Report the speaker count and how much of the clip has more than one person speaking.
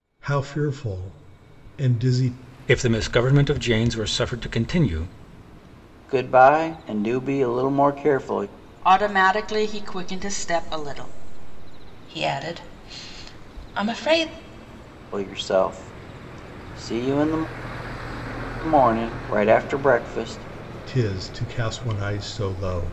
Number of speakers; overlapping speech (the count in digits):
5, no overlap